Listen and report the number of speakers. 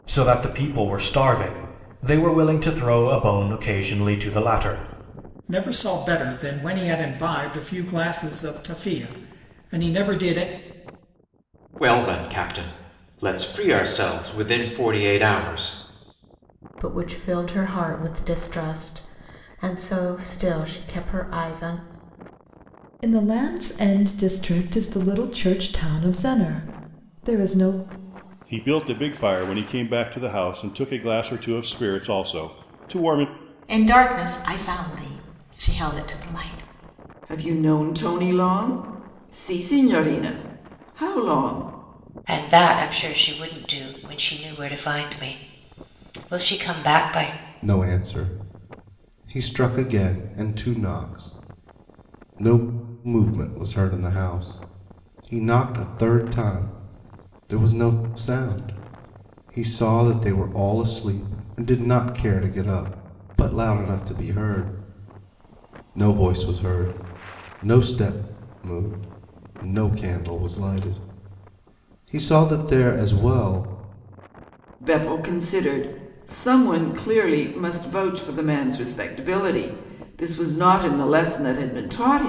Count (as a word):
ten